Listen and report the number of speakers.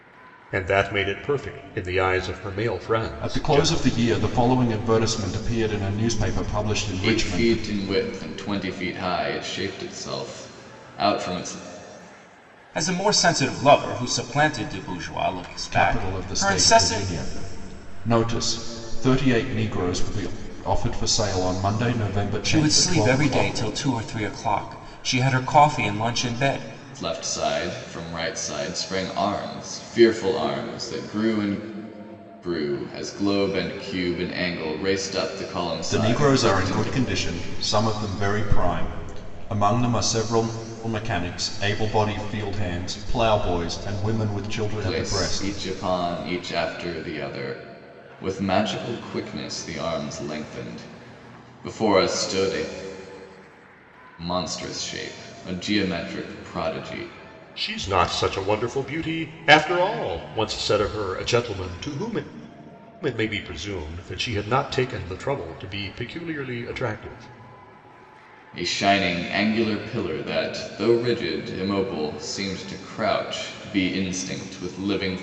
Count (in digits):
4